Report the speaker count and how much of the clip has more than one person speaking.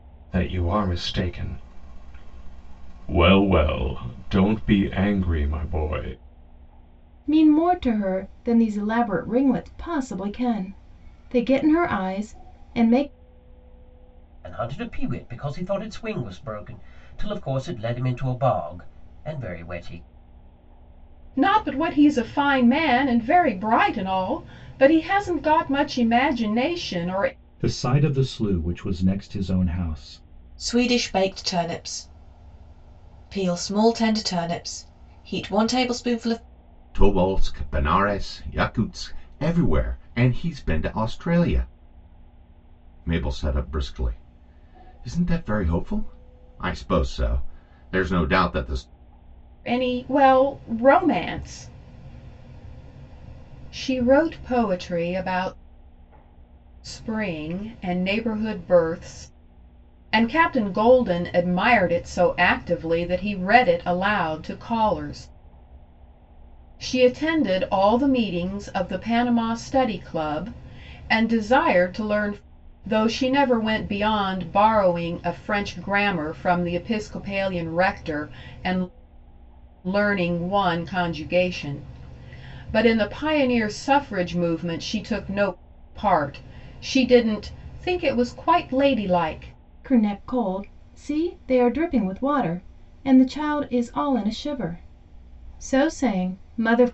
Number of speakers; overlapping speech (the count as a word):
seven, no overlap